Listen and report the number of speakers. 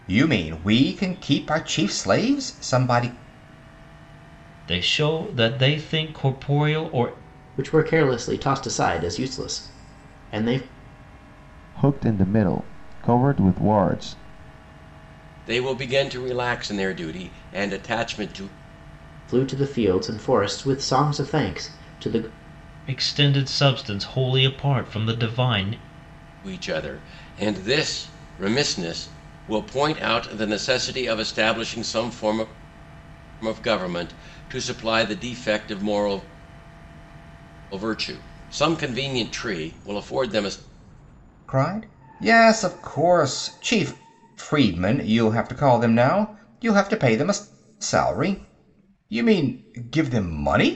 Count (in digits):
5